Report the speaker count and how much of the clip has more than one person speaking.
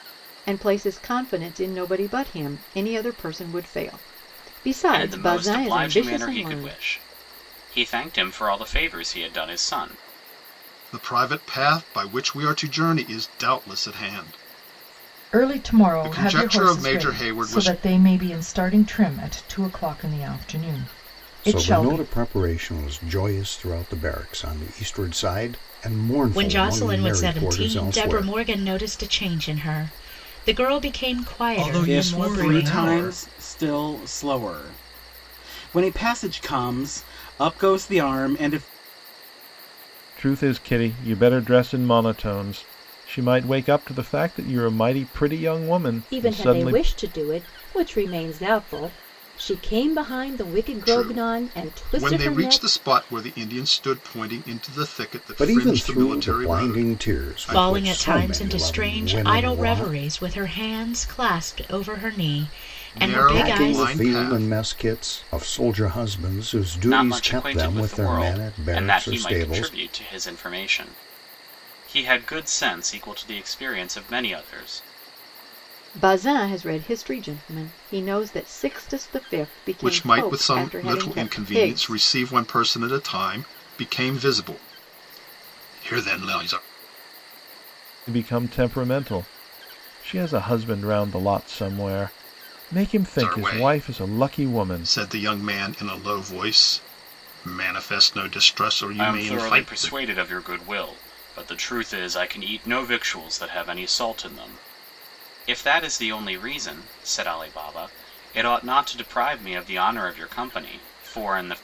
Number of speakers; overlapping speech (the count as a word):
ten, about 23%